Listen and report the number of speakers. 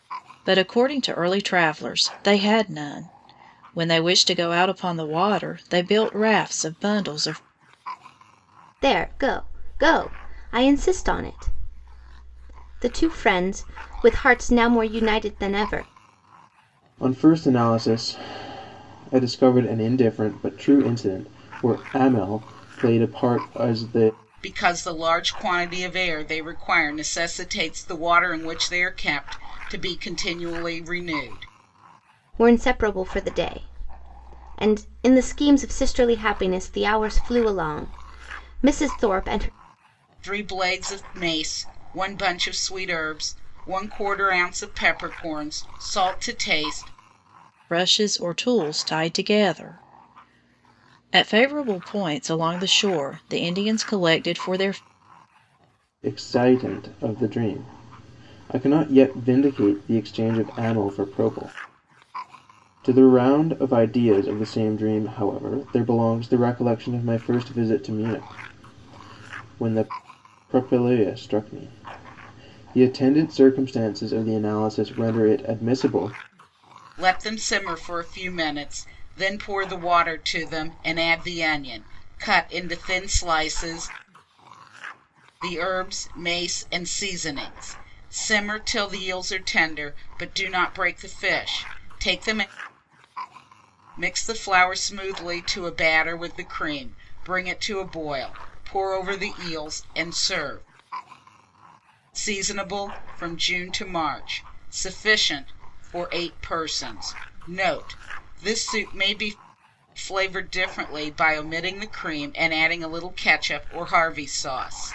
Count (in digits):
4